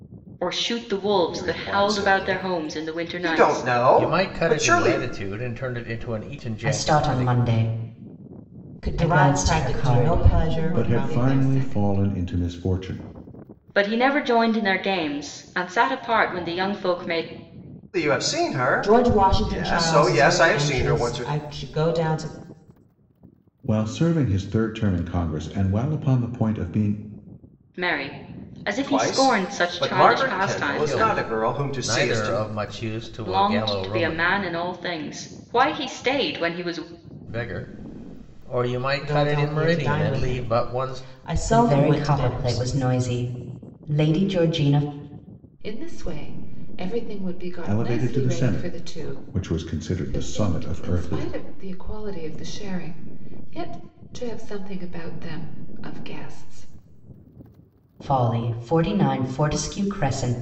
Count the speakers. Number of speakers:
seven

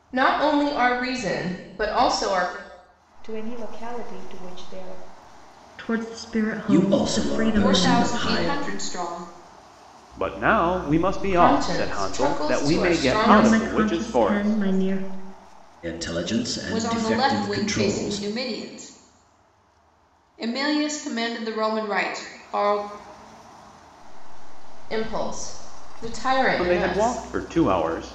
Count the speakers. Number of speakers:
seven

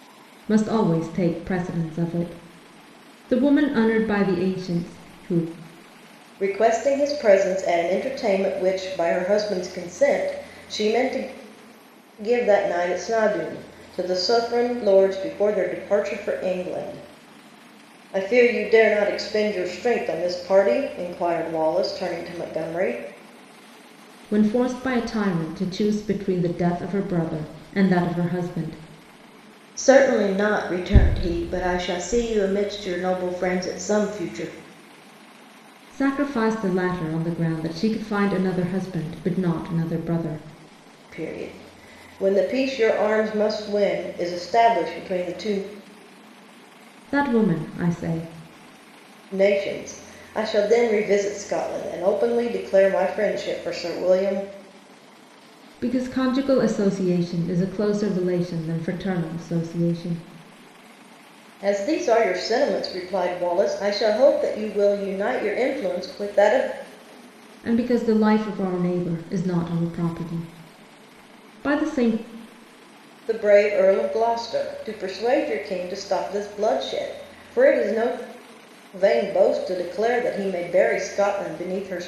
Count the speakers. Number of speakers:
two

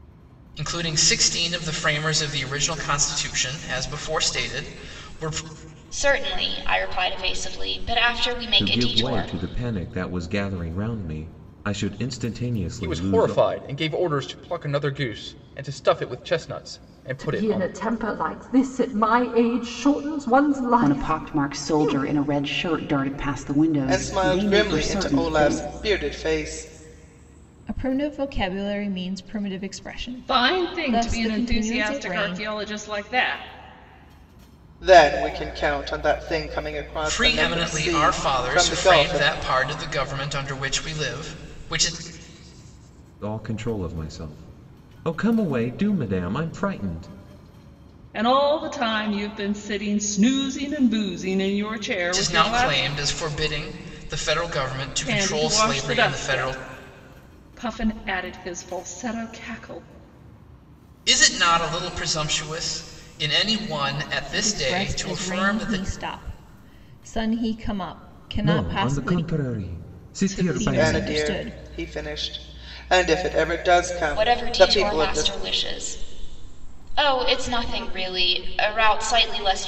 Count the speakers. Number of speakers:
nine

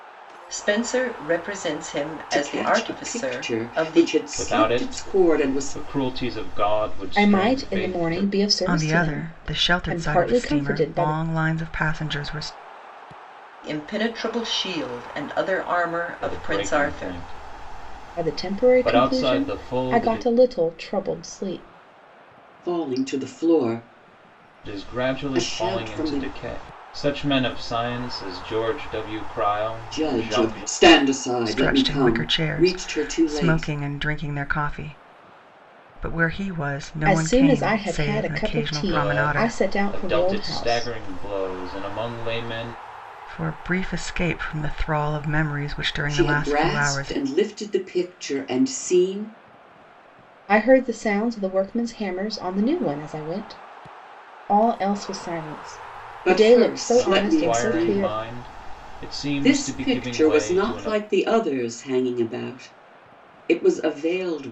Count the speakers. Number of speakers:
five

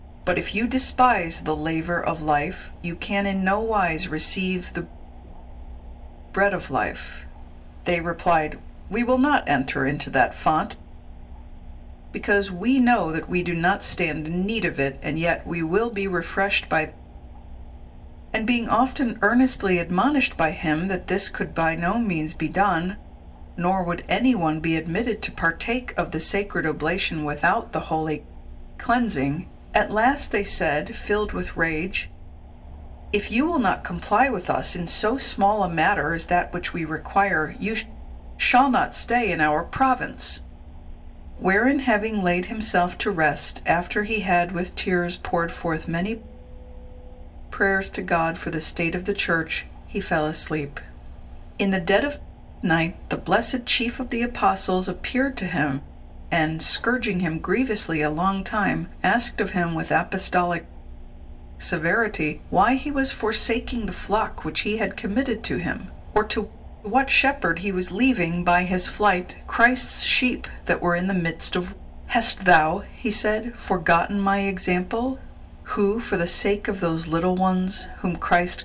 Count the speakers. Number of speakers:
one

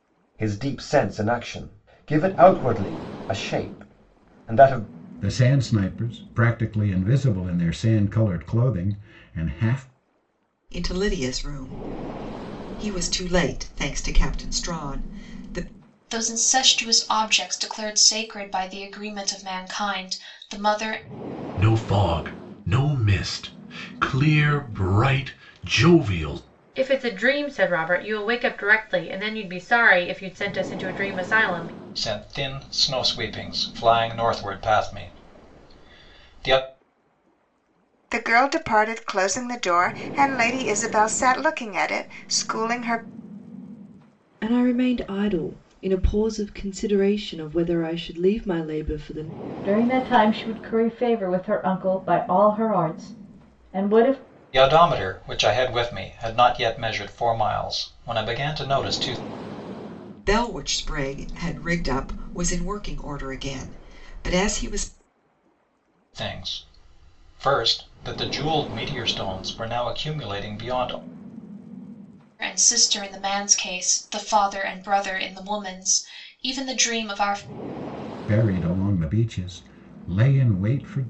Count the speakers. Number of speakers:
ten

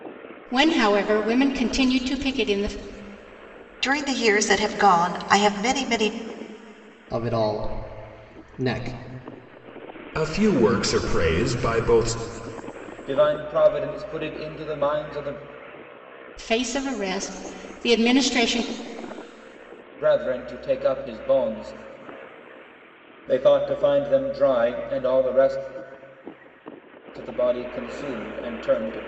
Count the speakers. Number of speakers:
five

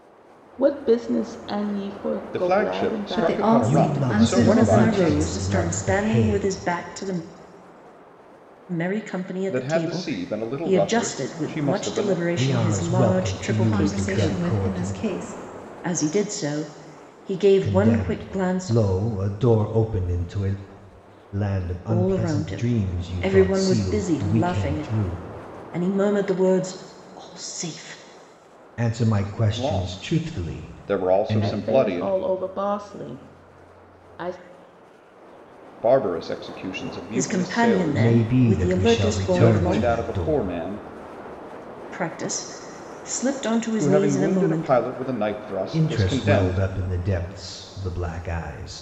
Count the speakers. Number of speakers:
five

